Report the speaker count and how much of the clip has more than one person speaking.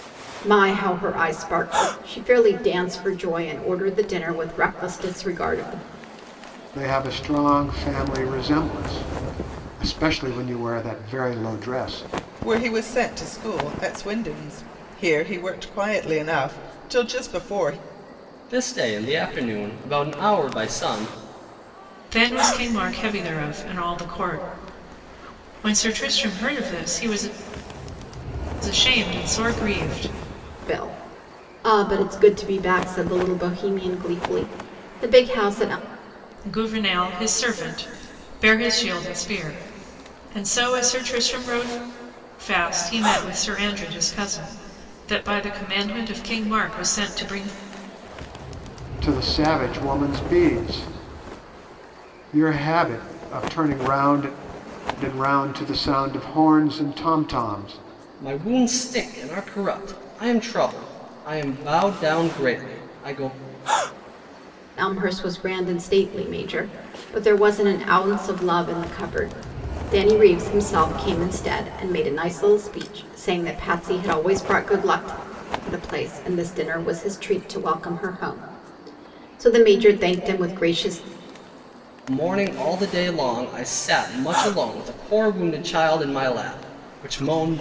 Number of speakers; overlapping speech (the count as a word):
five, no overlap